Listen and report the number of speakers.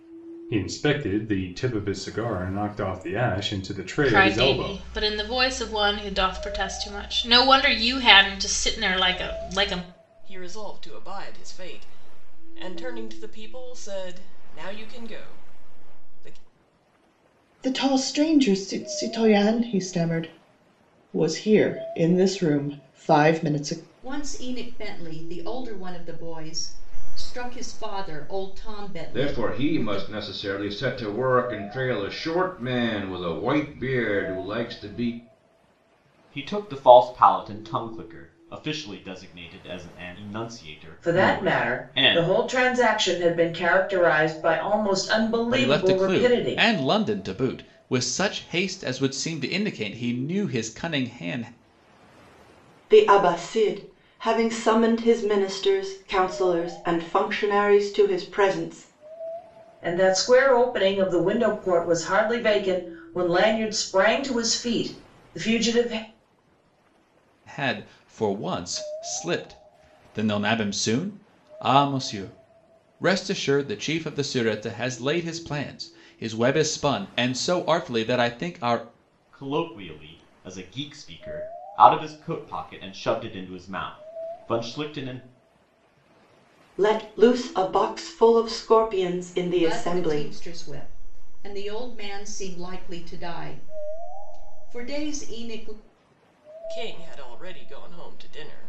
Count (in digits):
10